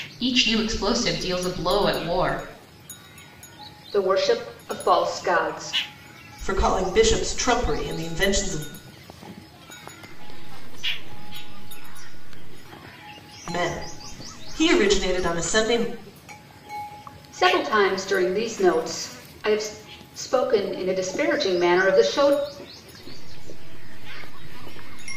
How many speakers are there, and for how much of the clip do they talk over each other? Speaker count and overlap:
four, no overlap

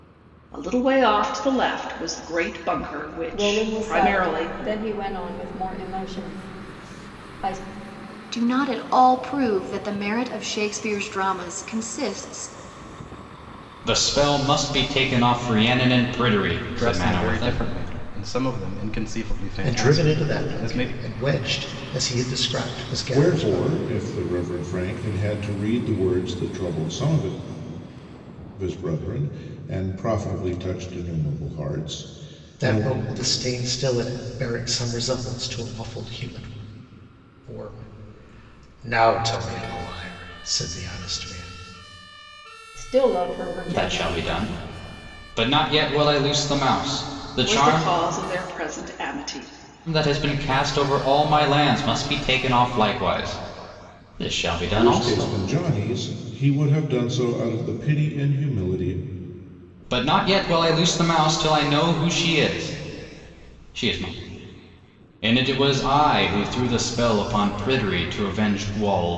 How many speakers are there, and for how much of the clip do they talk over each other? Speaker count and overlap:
seven, about 9%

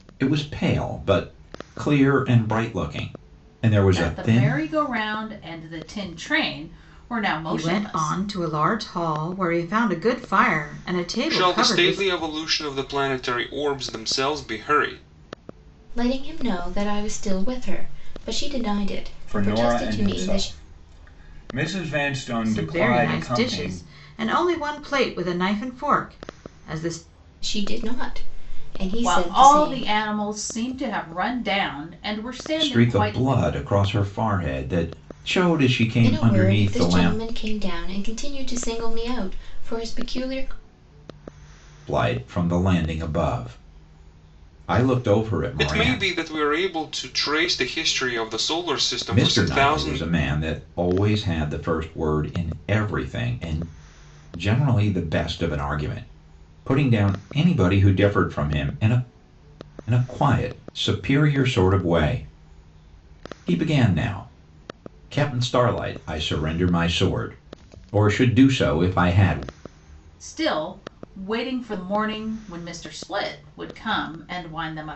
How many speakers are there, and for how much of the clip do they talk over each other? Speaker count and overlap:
six, about 12%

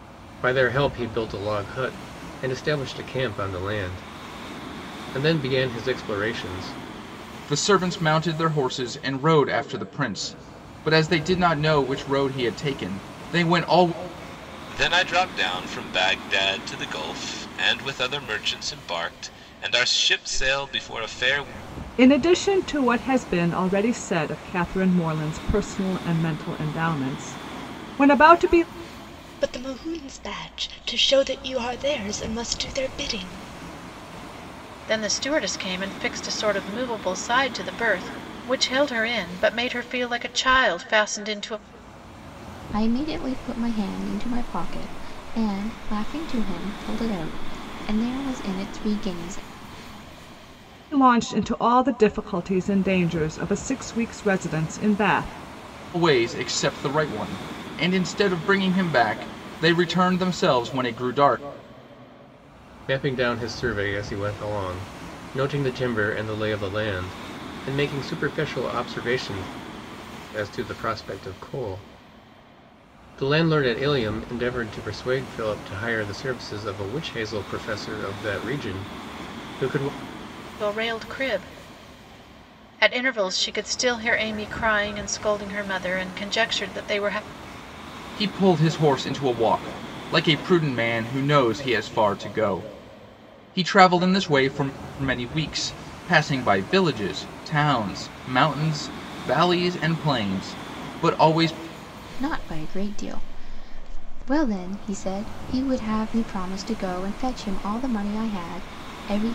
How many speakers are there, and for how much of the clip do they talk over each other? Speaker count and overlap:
seven, no overlap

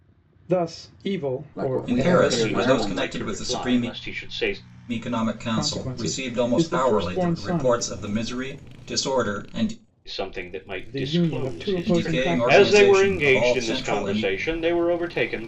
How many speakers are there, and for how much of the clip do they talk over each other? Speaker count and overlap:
four, about 53%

